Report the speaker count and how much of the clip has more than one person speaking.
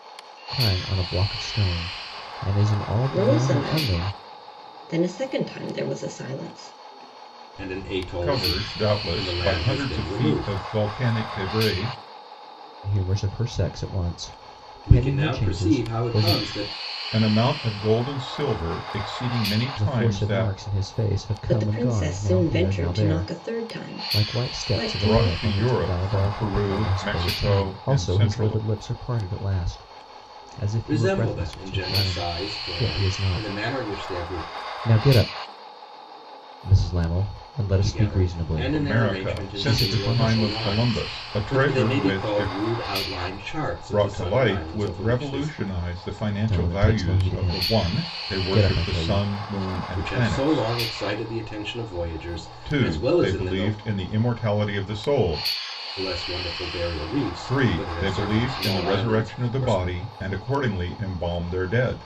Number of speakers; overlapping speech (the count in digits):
4, about 48%